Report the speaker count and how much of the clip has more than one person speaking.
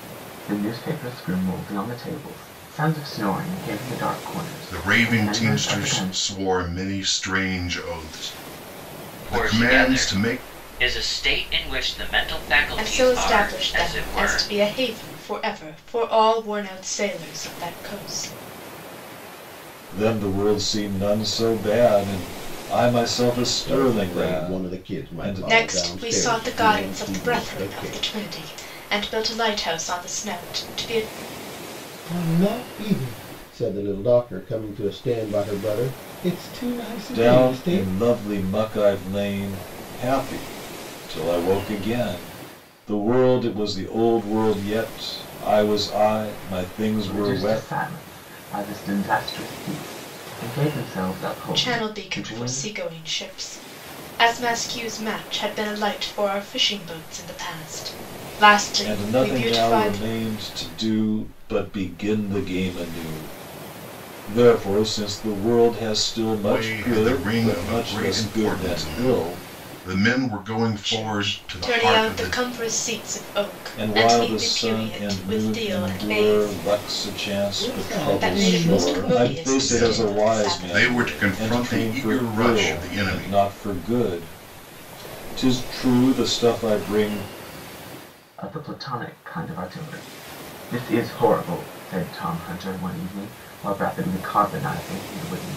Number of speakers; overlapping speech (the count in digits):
6, about 28%